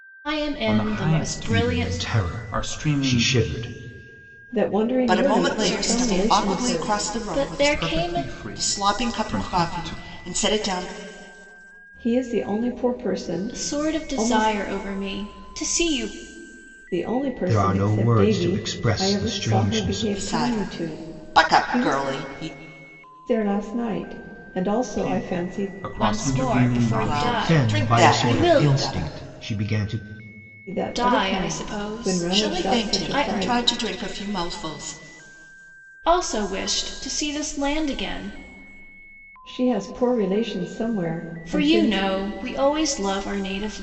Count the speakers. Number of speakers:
five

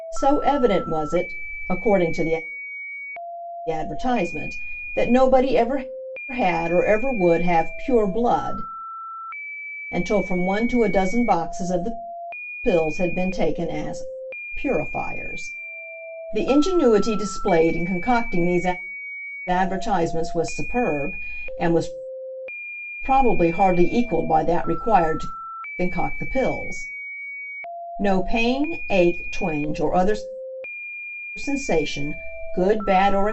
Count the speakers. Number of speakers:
one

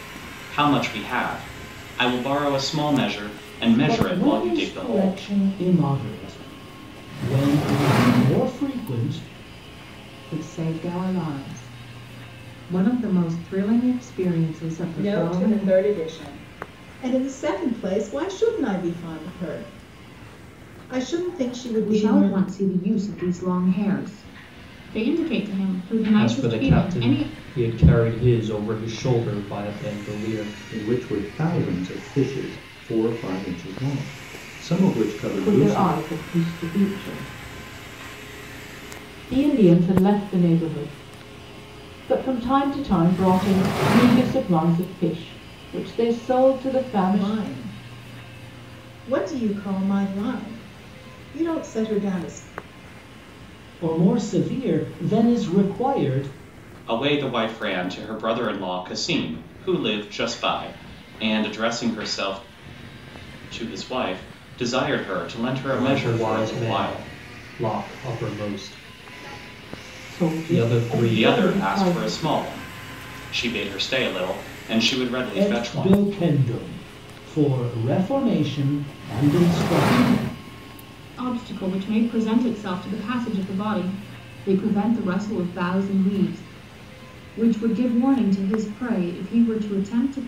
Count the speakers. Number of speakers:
nine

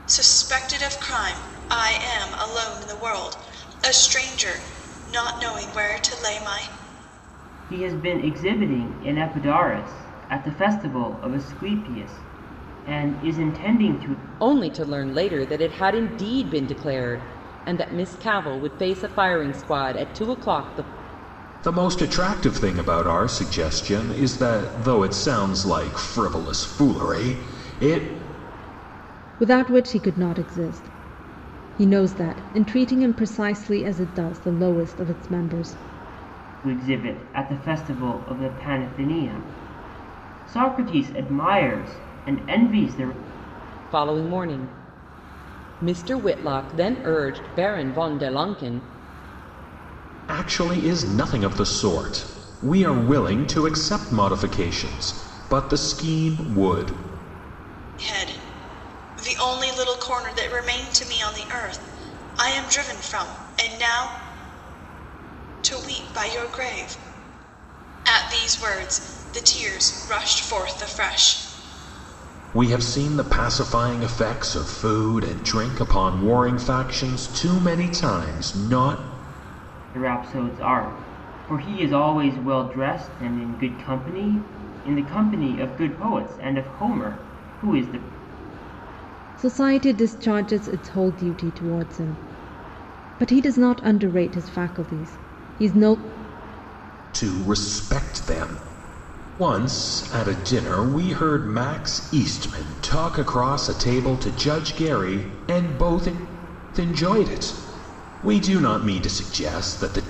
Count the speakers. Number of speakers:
five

